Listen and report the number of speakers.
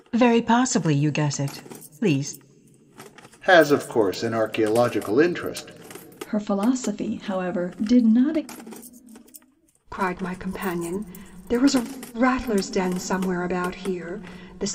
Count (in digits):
4